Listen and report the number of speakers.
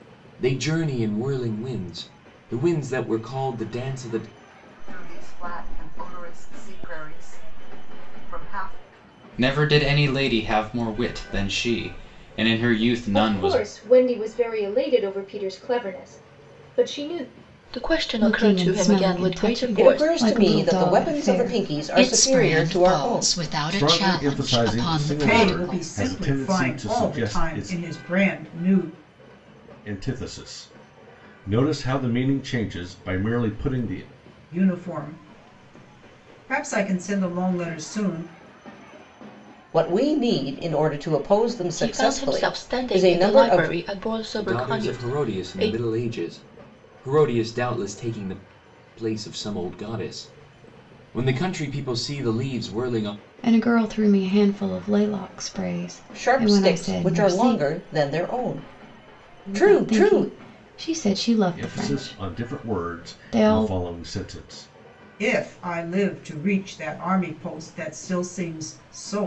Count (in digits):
10